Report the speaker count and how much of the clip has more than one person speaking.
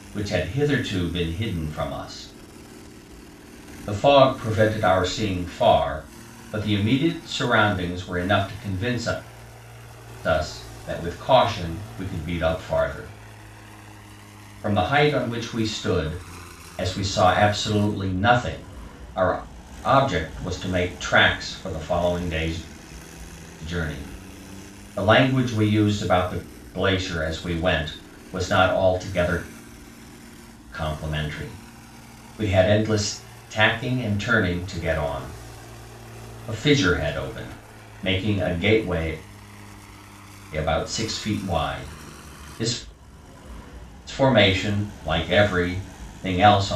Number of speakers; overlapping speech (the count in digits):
1, no overlap